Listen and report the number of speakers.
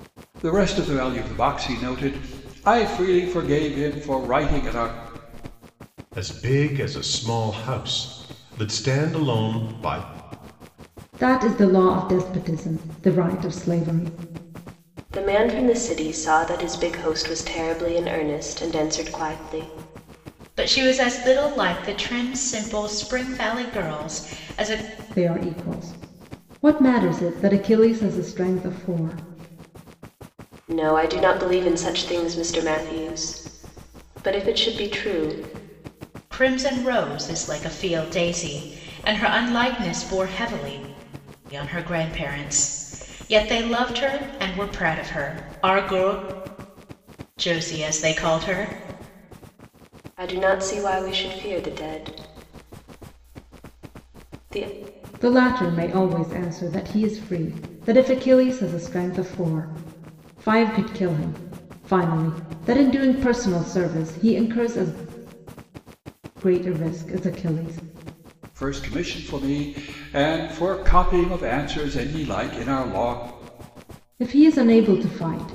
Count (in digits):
5